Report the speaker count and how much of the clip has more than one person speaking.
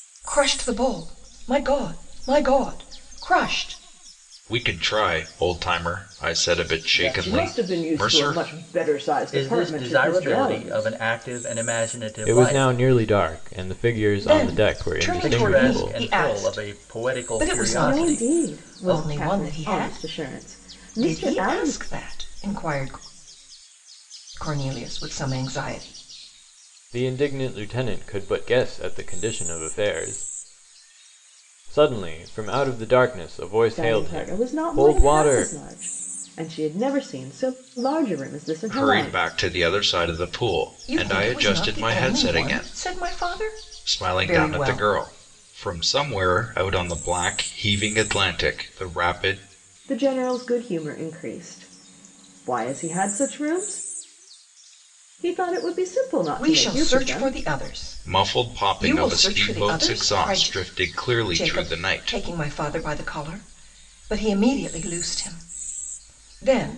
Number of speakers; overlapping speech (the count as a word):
five, about 32%